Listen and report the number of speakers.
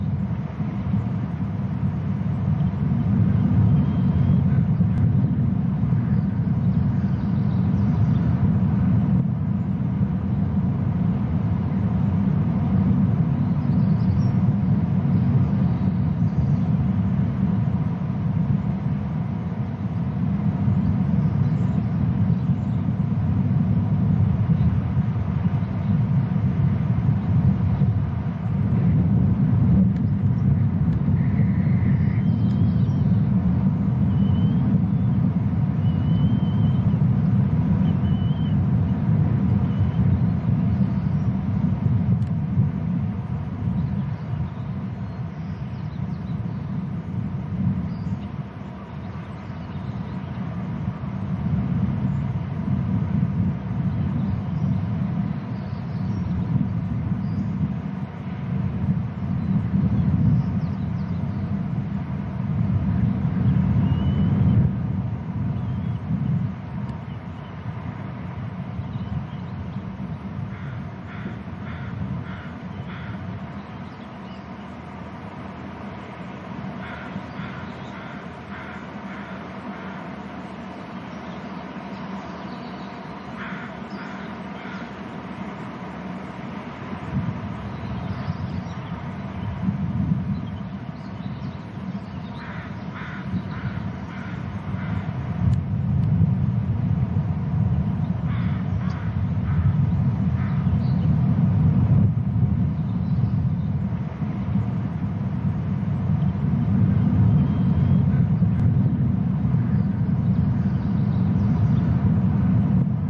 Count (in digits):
0